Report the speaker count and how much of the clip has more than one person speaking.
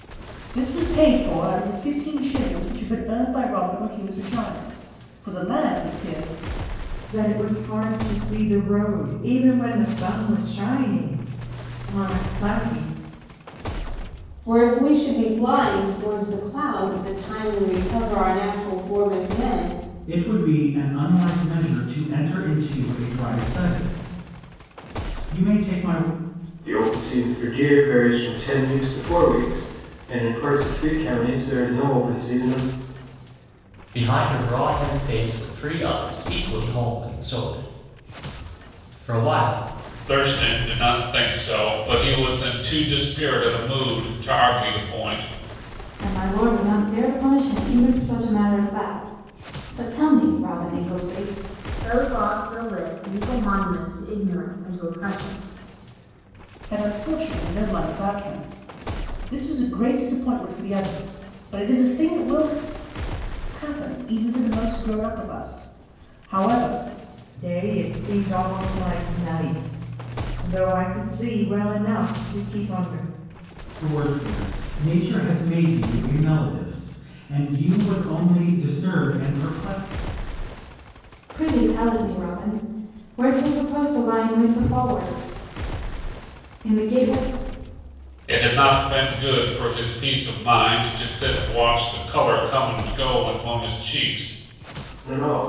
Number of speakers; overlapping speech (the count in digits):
9, no overlap